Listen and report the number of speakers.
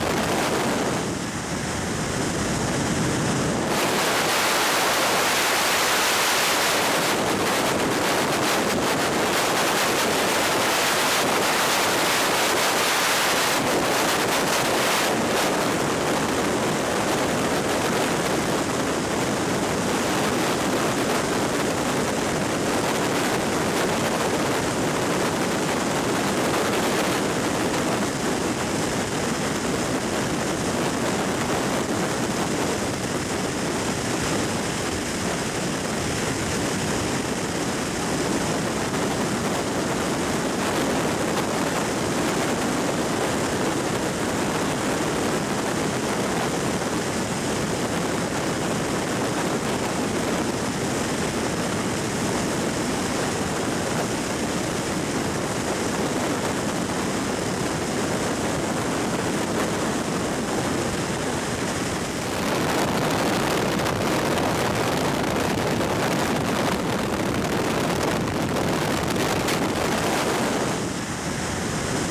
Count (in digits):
0